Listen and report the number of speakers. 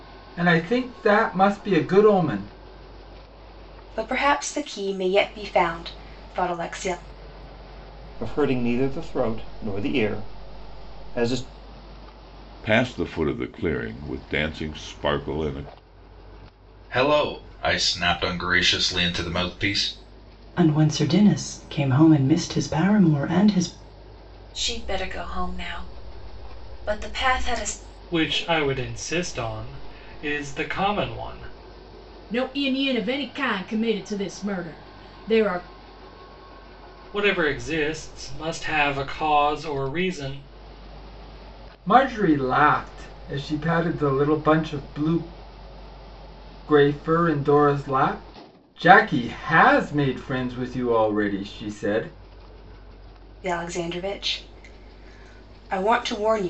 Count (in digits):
9